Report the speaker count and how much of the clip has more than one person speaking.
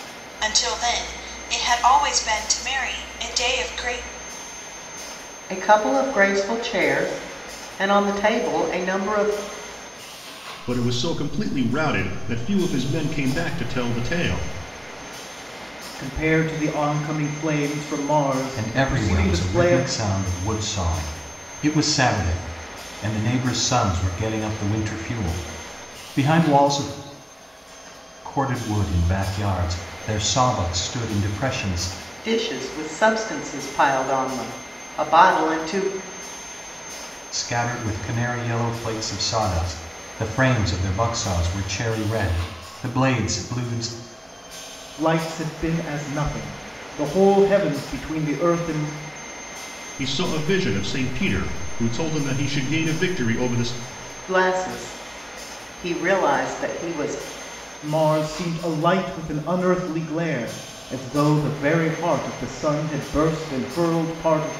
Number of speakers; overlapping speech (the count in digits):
5, about 2%